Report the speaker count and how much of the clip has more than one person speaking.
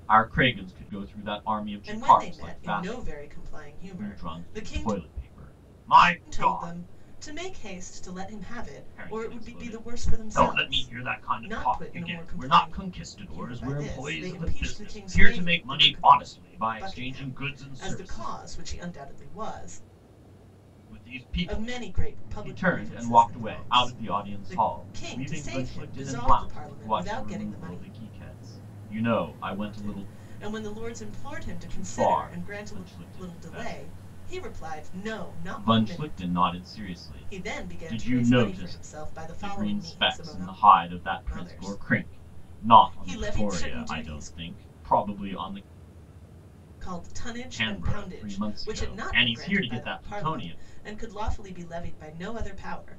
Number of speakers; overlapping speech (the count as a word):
two, about 56%